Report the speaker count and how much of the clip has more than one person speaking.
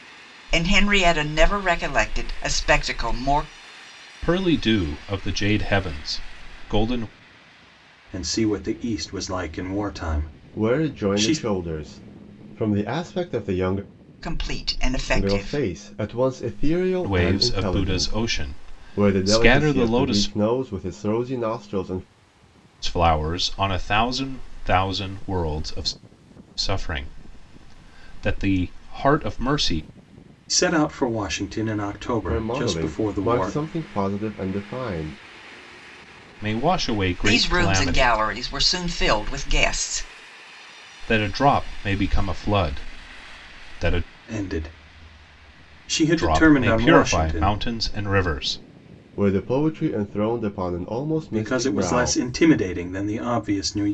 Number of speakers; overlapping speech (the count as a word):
four, about 16%